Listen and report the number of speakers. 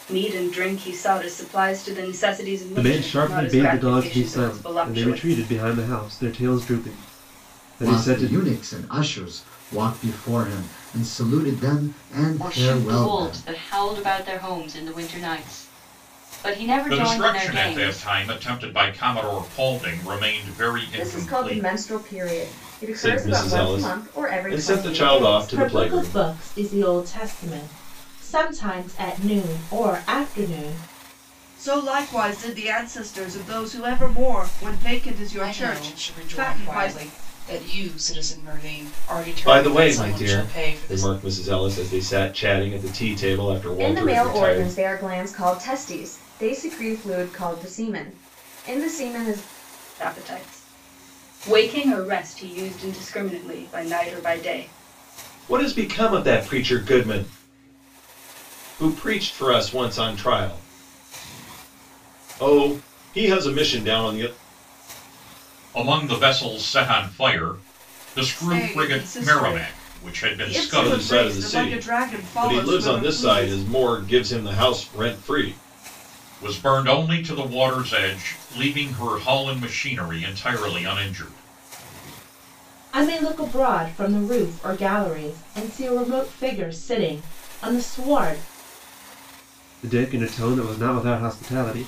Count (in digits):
10